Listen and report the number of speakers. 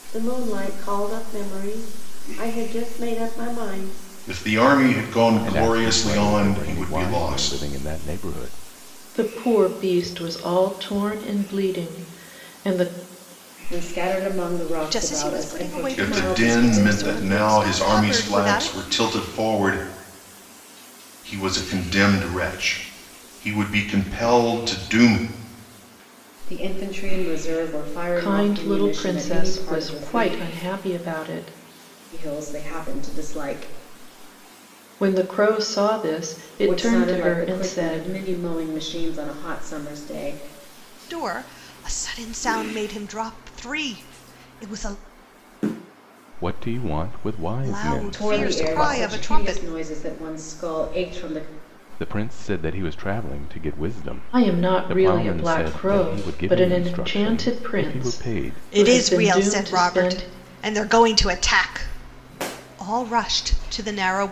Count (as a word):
six